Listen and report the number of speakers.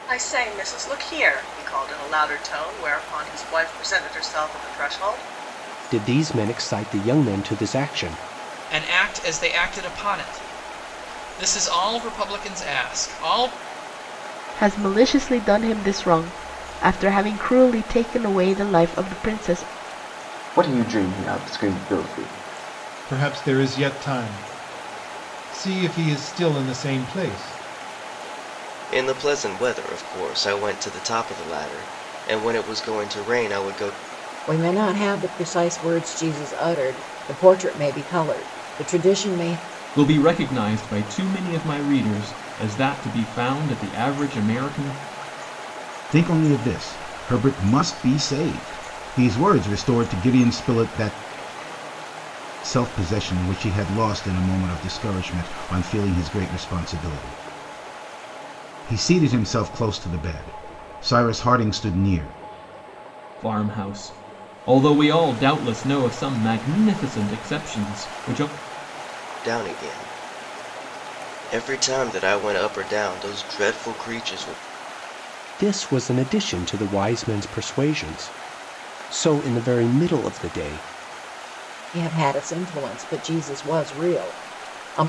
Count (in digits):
10